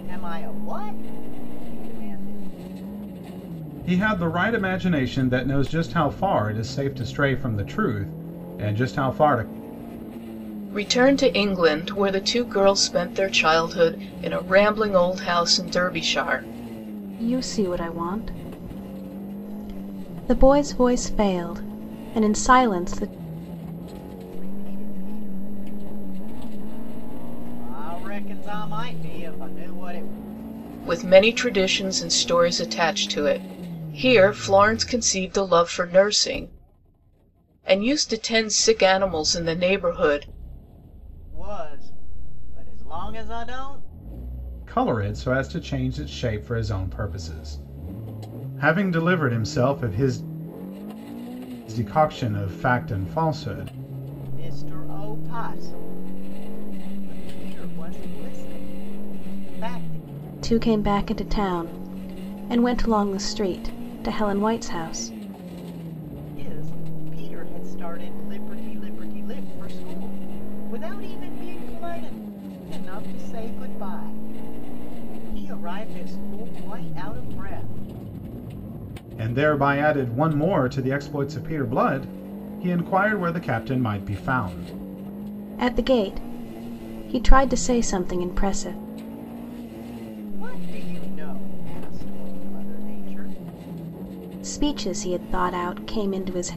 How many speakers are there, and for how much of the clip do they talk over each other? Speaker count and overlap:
4, no overlap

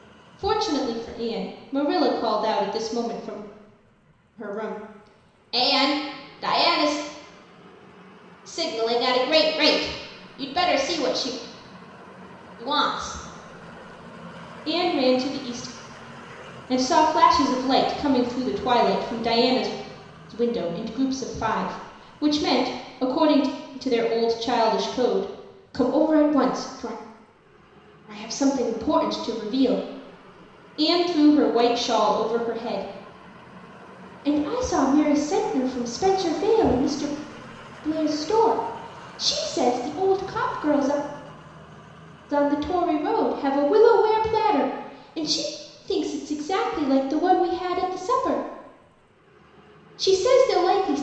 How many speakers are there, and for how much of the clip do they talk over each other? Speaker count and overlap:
1, no overlap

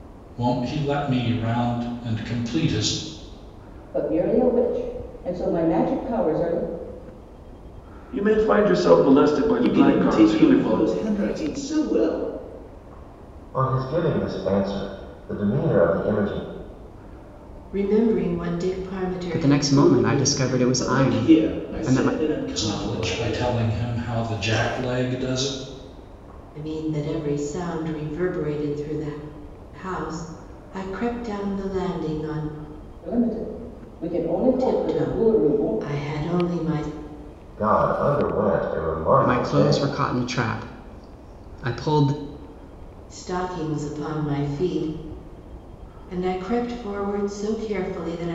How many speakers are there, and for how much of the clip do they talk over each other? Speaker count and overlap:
7, about 15%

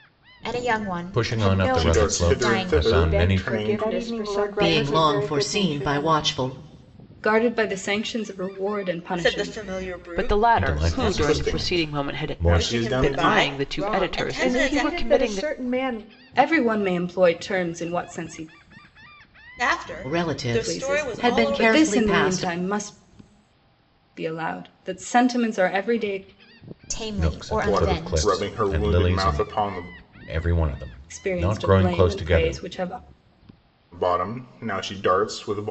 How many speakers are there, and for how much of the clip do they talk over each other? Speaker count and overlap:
9, about 49%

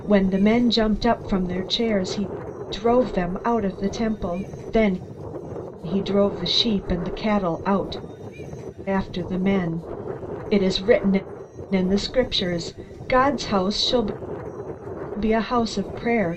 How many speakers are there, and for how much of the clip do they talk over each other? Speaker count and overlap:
1, no overlap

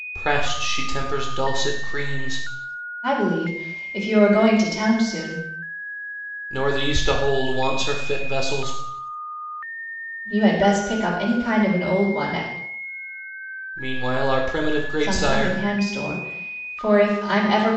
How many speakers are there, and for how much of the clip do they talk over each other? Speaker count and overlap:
2, about 4%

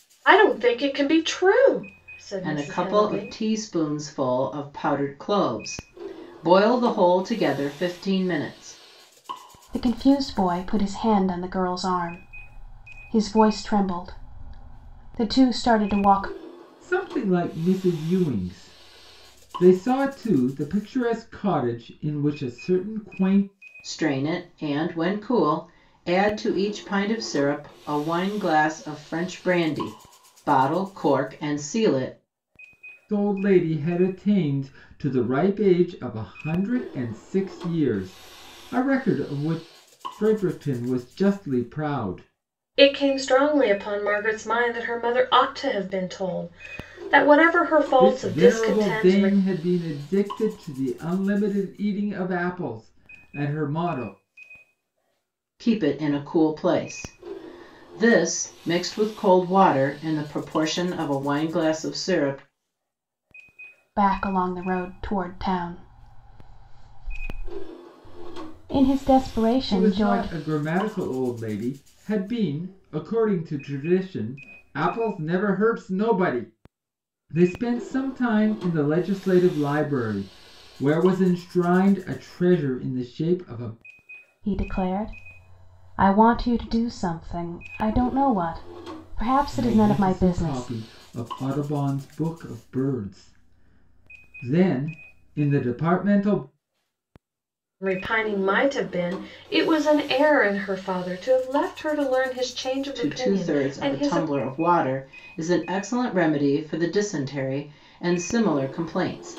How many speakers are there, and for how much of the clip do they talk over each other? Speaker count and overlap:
4, about 5%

